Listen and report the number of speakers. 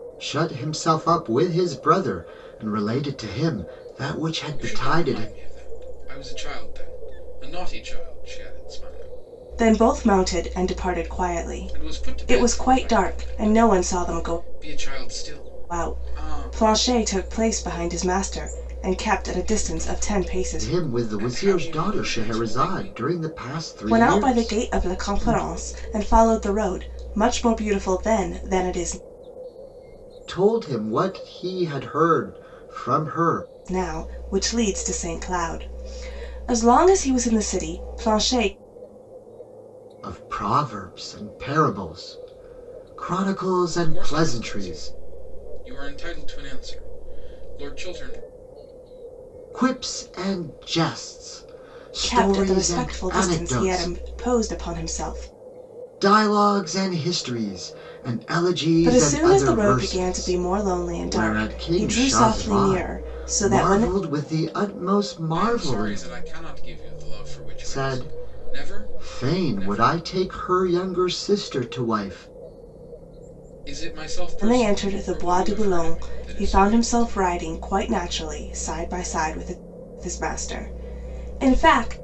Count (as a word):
three